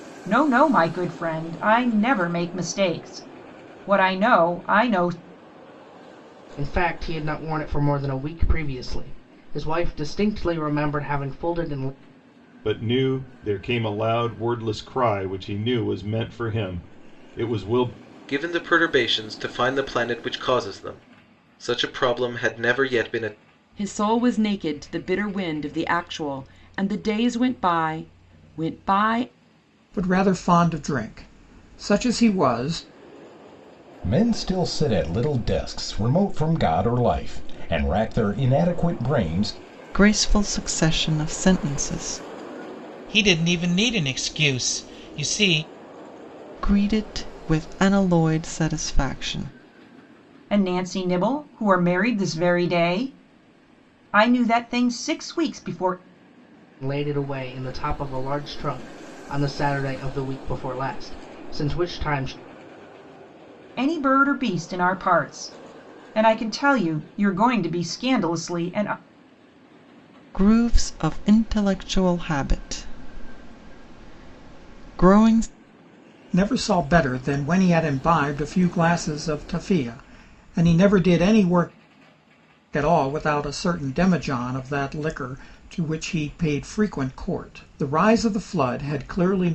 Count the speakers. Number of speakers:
9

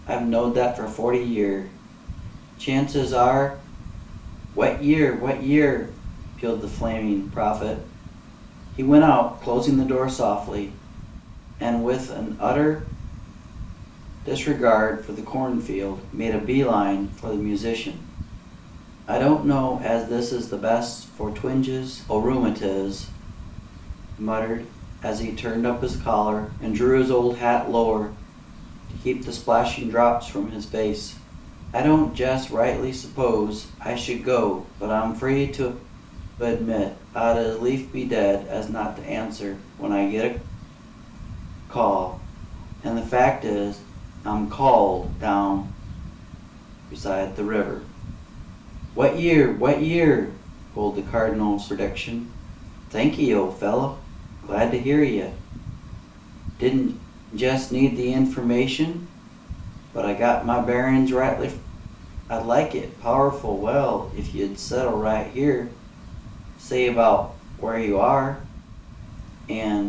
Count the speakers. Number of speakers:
1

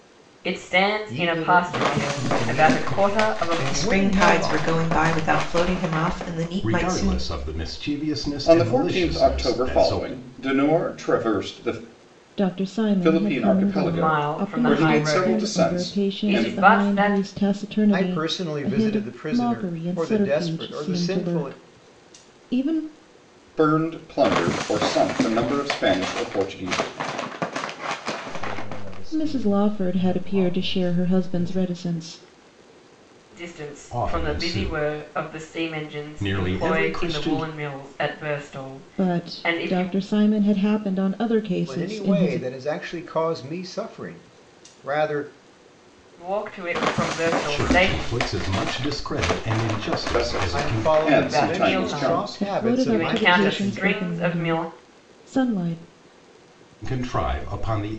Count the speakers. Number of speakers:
7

